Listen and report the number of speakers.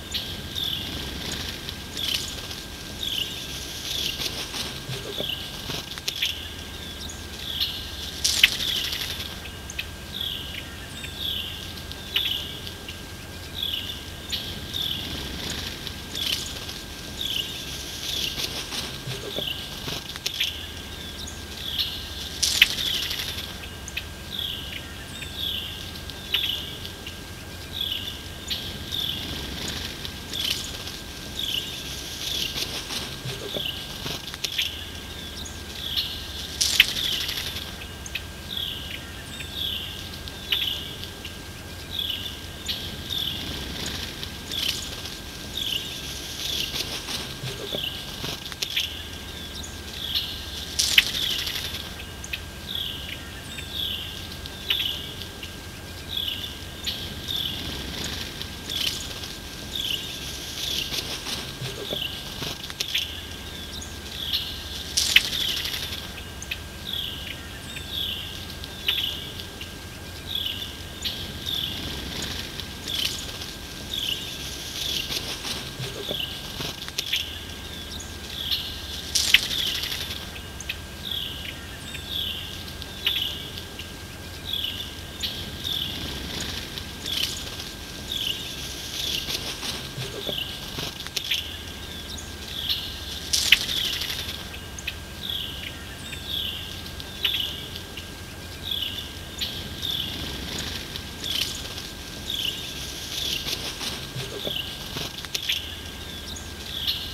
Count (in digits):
0